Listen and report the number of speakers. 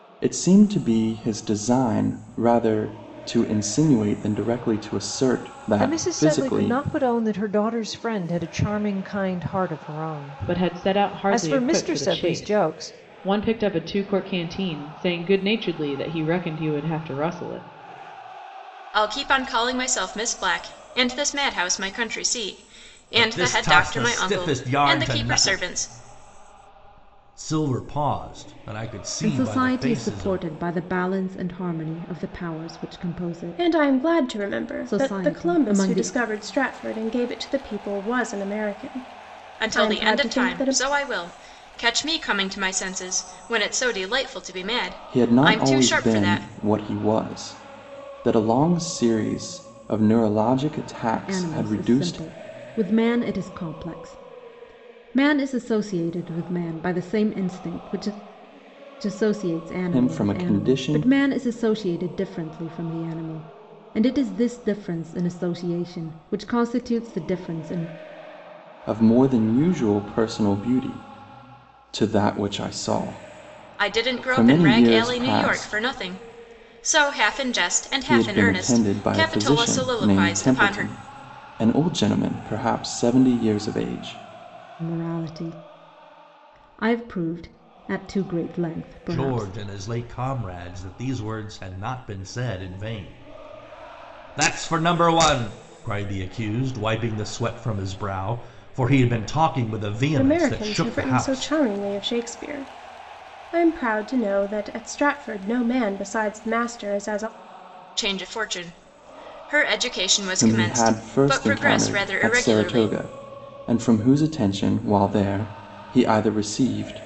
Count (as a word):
seven